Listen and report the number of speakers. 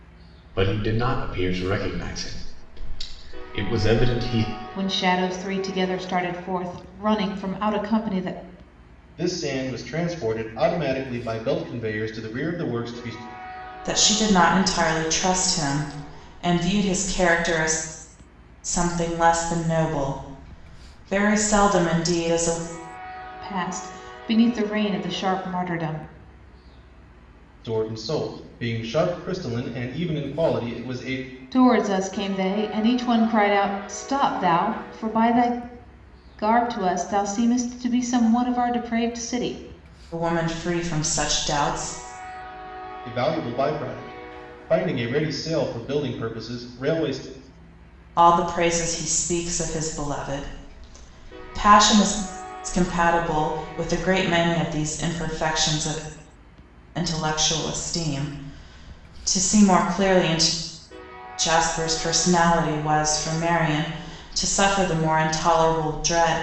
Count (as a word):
four